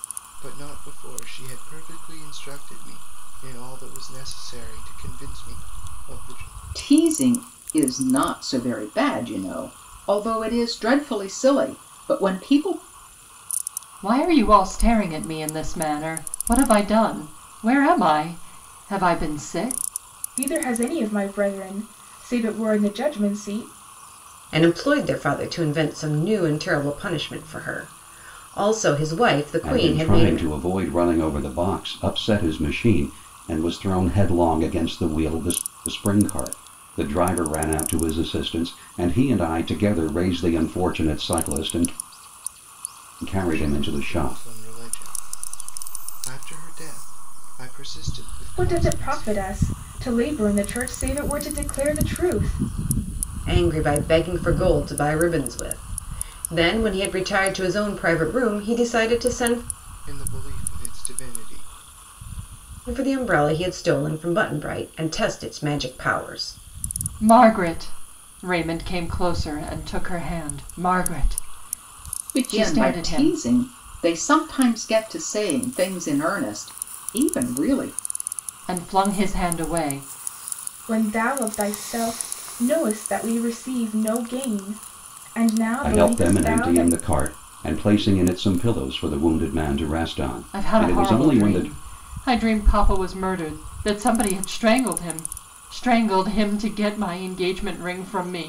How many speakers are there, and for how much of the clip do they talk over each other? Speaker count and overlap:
six, about 6%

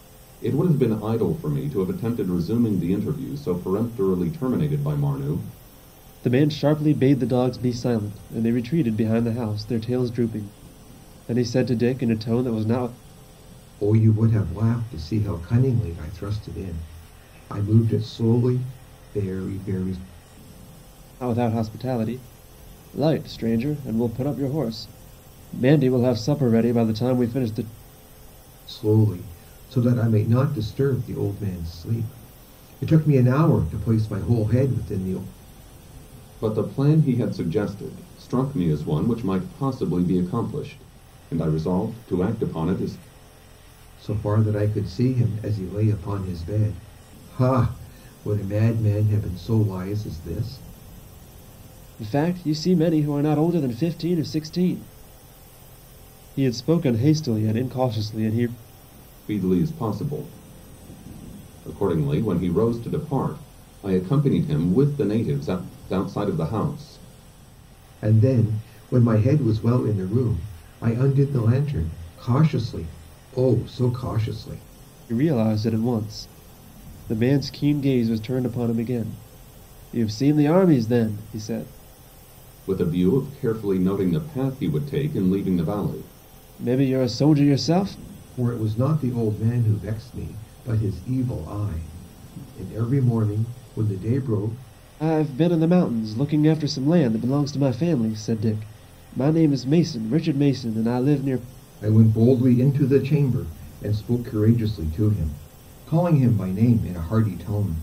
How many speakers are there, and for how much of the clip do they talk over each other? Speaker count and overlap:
three, no overlap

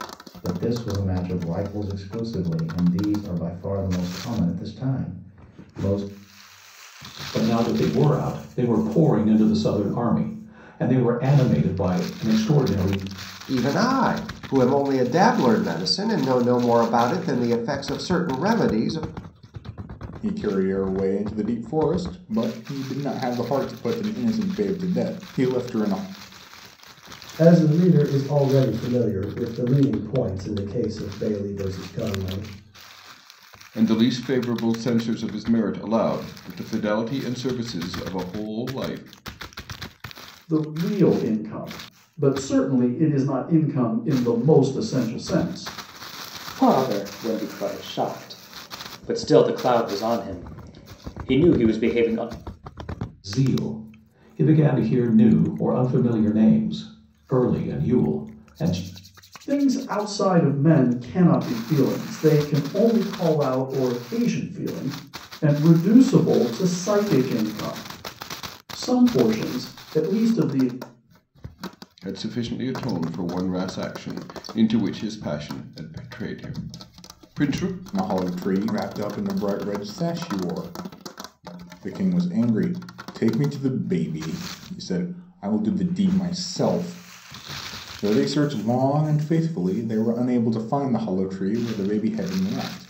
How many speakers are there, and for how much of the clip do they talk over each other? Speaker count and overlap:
eight, no overlap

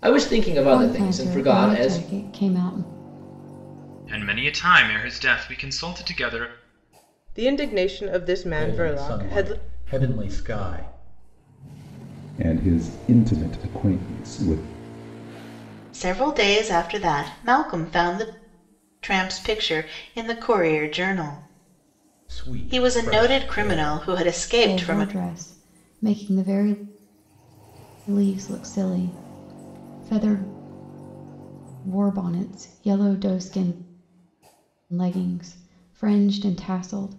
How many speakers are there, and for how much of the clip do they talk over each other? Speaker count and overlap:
seven, about 12%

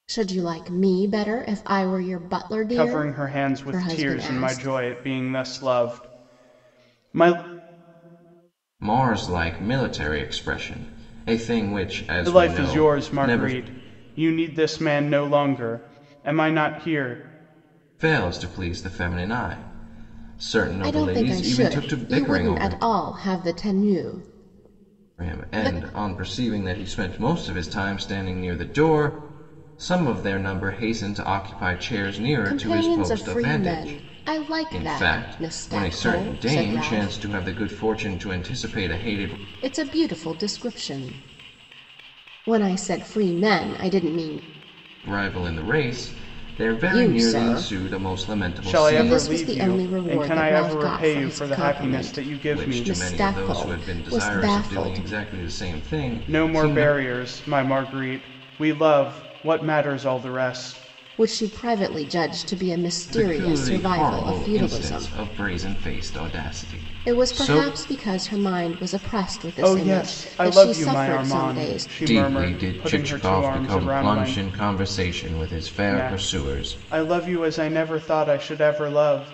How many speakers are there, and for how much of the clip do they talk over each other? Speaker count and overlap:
three, about 34%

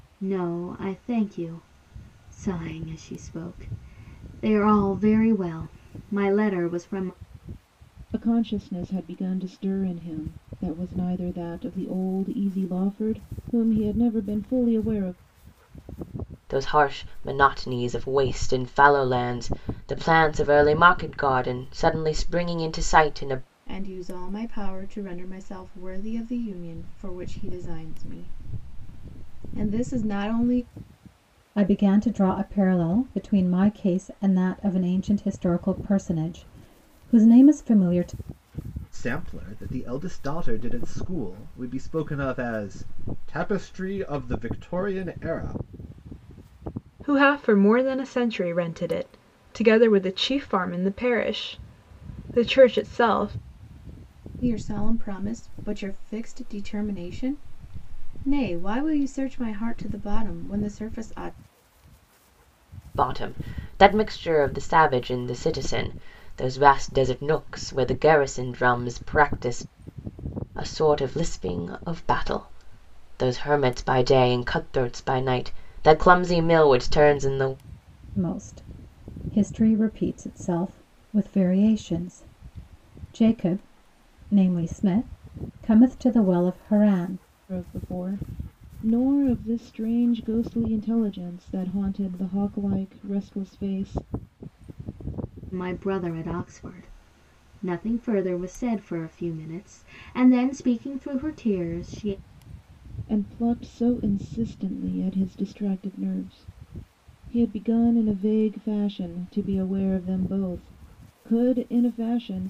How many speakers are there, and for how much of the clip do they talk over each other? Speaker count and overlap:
seven, no overlap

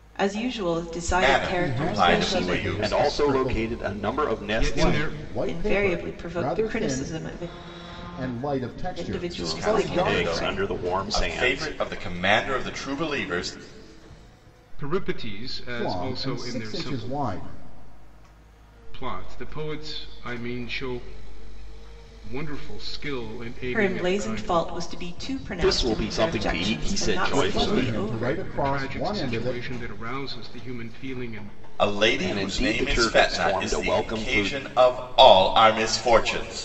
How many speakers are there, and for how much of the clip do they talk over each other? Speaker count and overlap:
five, about 45%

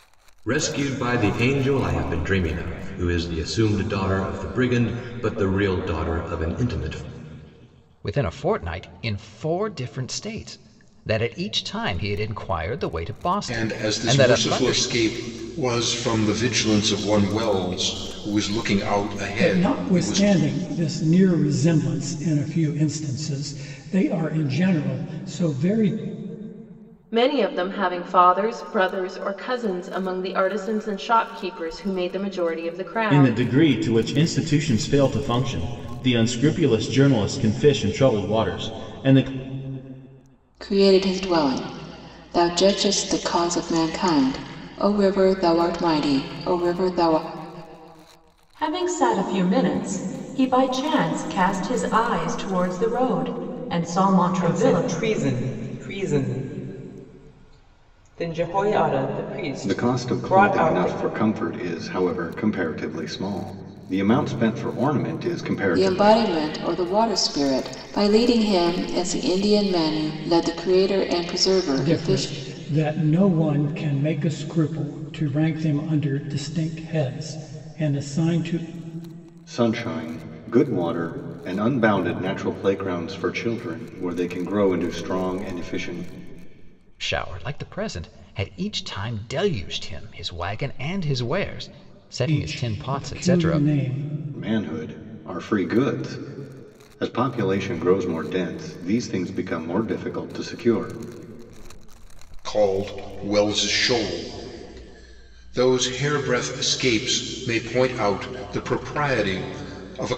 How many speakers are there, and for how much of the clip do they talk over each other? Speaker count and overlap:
ten, about 6%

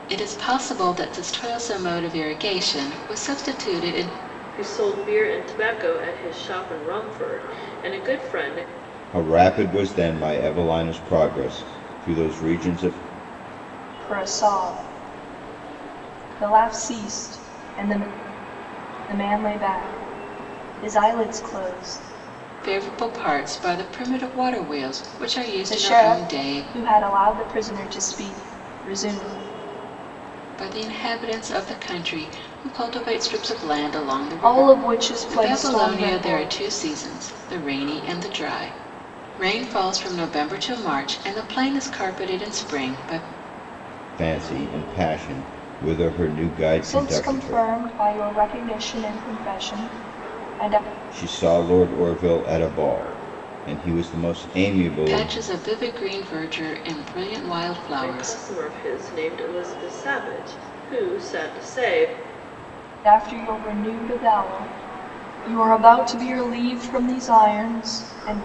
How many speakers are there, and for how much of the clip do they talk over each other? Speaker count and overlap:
four, about 6%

